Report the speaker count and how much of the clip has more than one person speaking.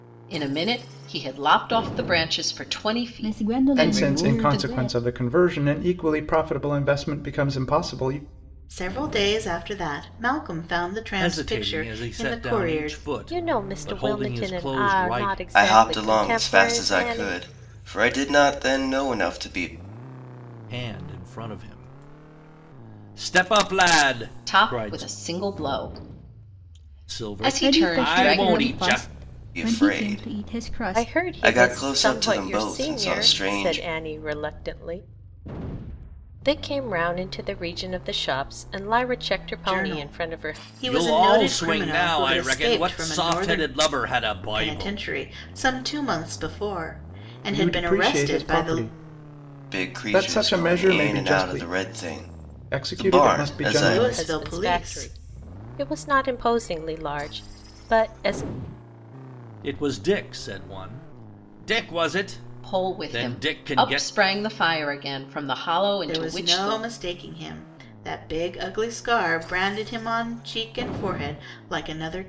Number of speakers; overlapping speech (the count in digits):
7, about 38%